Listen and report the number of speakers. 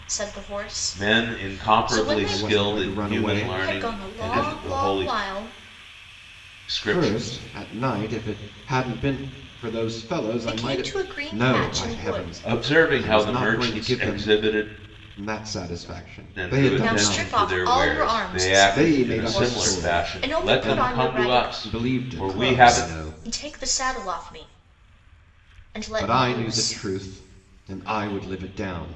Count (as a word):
three